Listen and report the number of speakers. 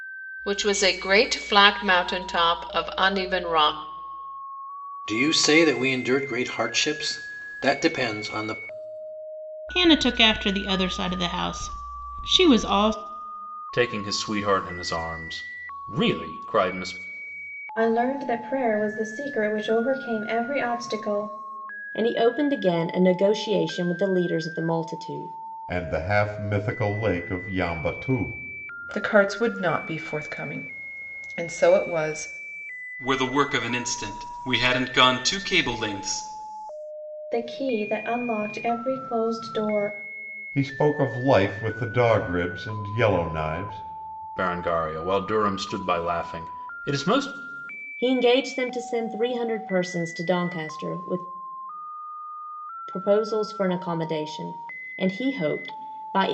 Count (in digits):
9